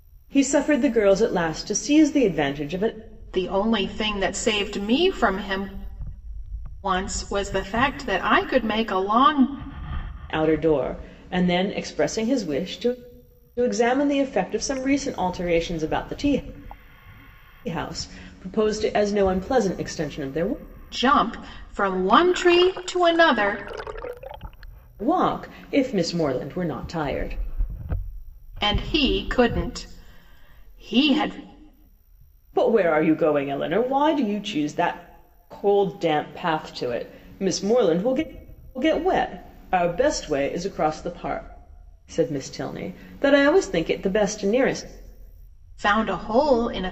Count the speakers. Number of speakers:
2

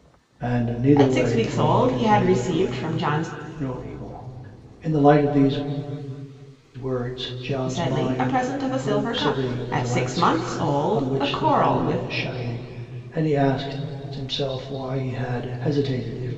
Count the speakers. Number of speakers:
2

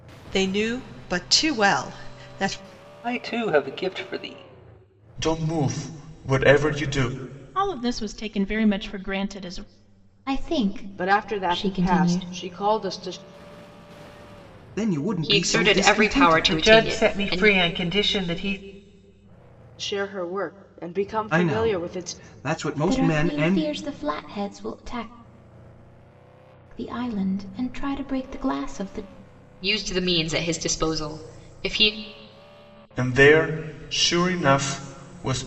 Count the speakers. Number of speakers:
9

